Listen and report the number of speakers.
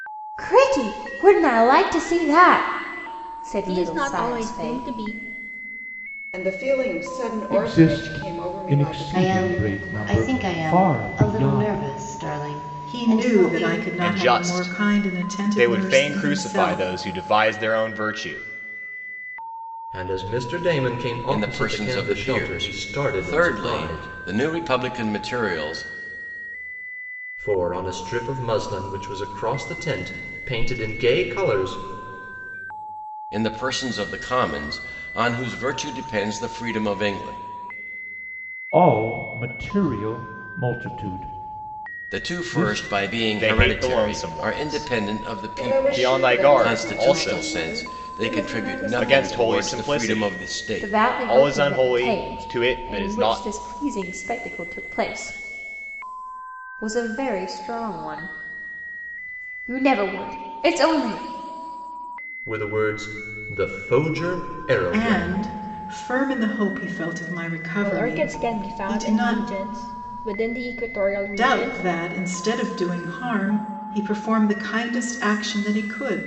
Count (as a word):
nine